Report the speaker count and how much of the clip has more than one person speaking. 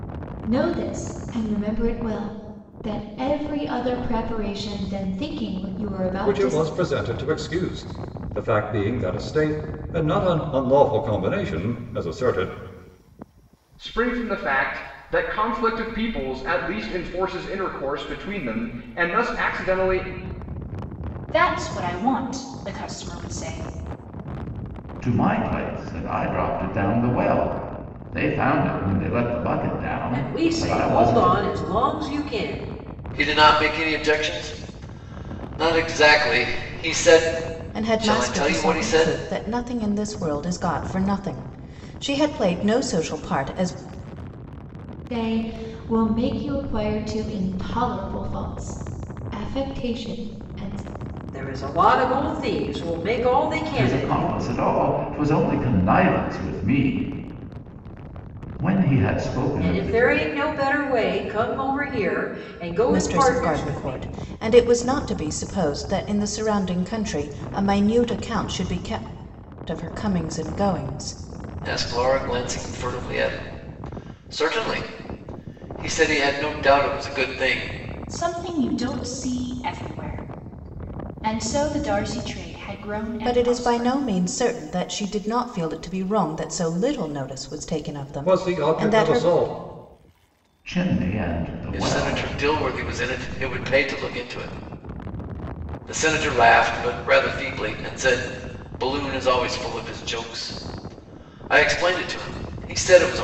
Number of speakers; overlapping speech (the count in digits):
8, about 8%